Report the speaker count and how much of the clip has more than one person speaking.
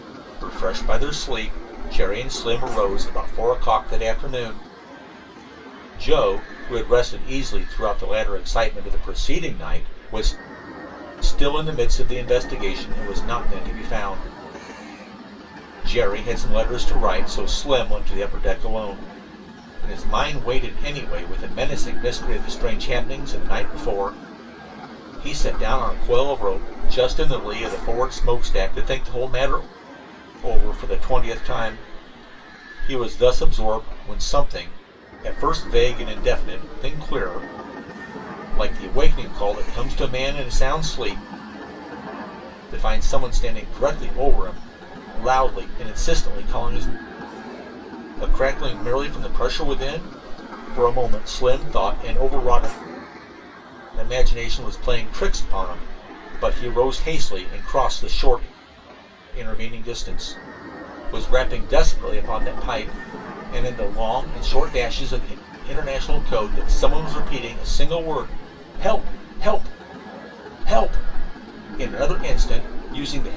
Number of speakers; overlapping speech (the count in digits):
1, no overlap